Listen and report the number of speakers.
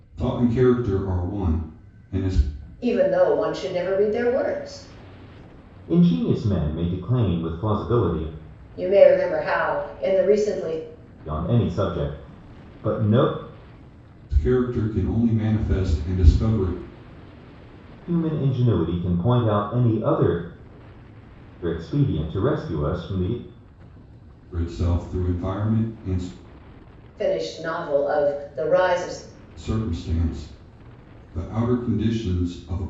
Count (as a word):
three